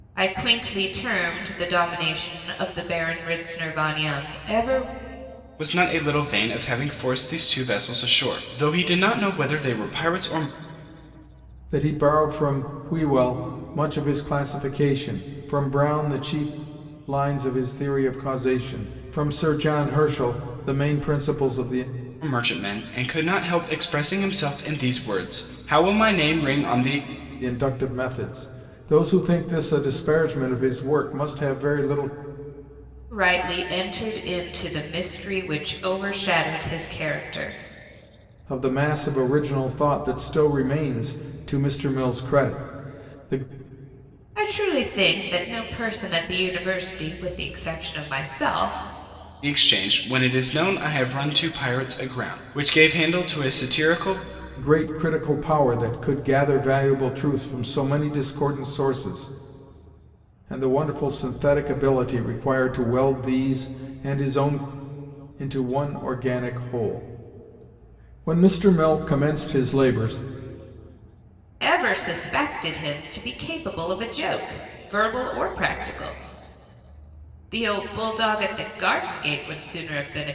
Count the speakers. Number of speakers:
3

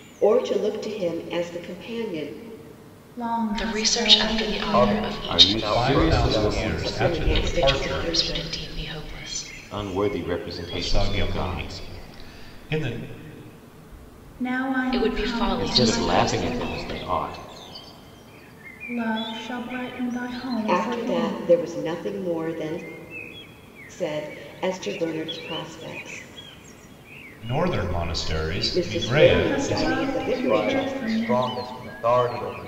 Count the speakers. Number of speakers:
6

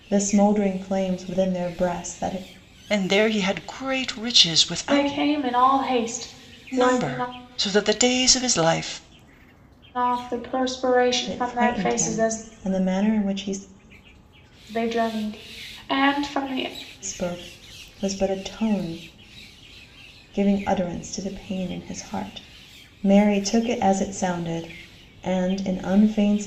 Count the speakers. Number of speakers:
3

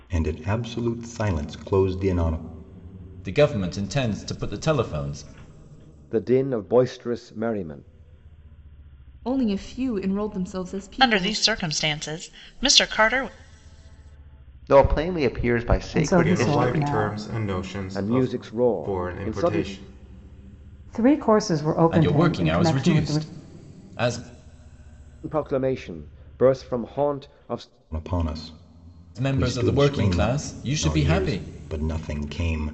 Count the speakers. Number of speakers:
8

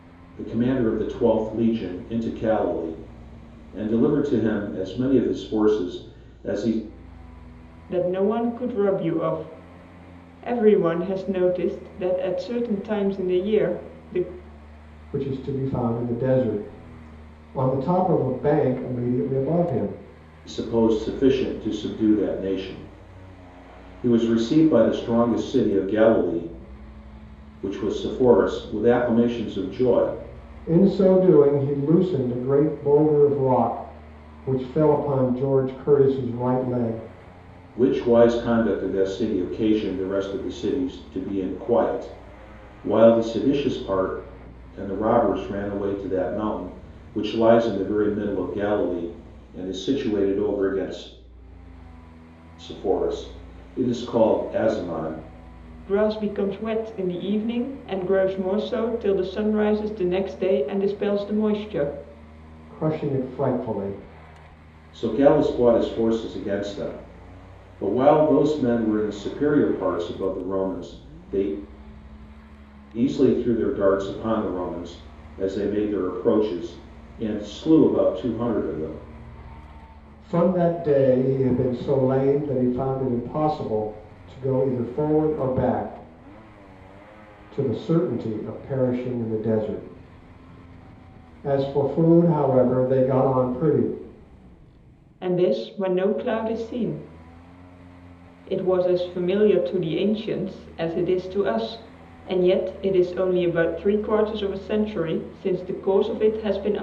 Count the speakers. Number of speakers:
3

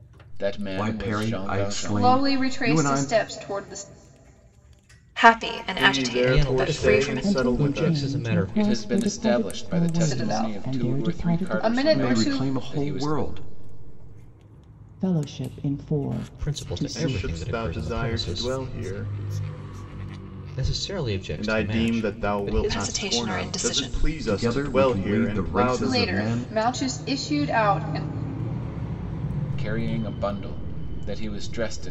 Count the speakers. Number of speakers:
7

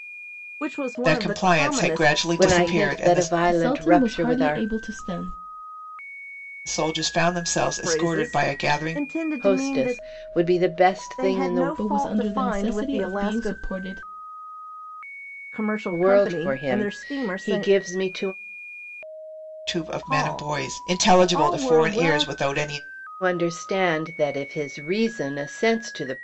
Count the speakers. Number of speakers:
4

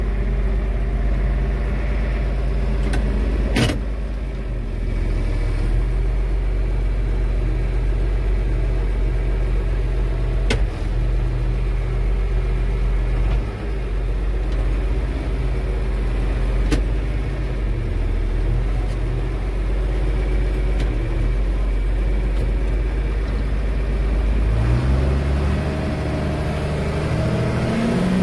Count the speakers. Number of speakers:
0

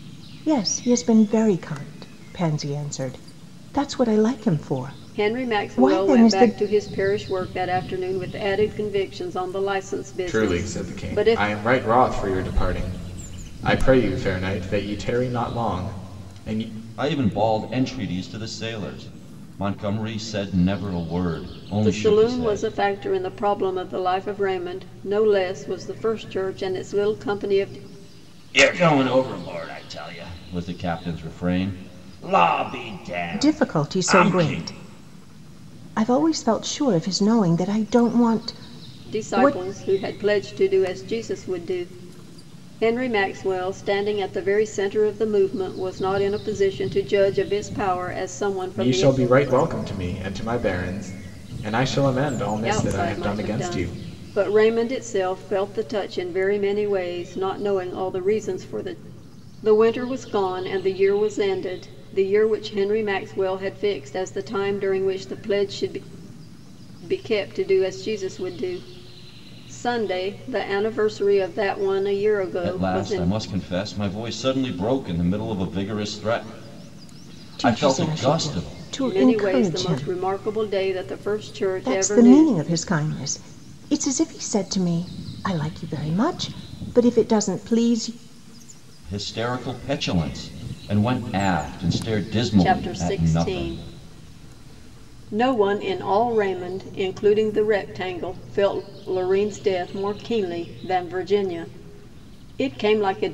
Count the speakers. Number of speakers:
4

